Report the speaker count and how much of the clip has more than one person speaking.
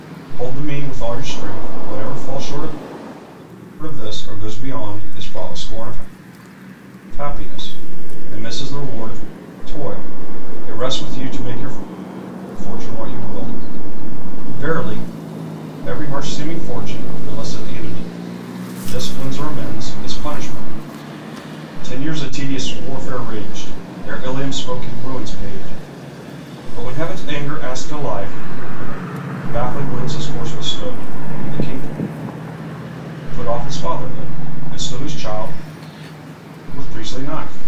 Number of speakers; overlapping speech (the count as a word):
one, no overlap